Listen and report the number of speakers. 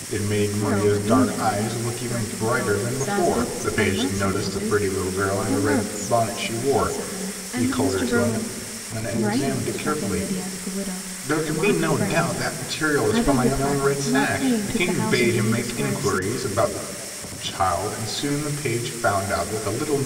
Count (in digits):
2